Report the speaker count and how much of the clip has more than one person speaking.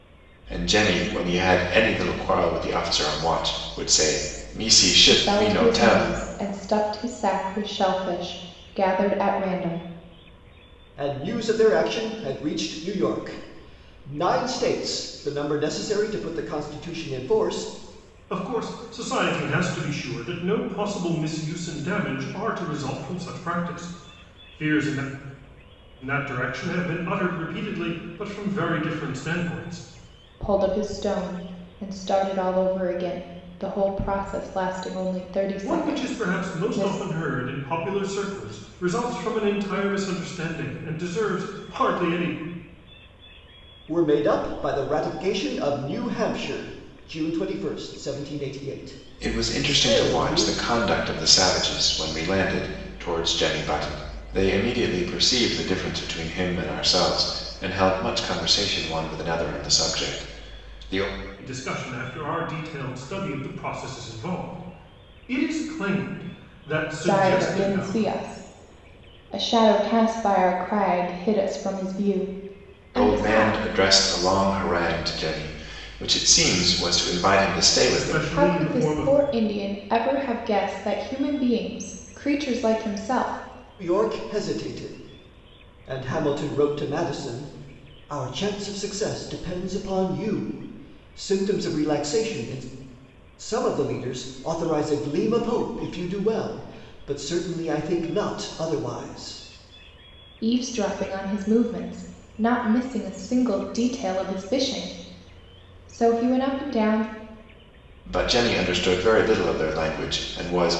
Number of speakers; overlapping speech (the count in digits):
4, about 6%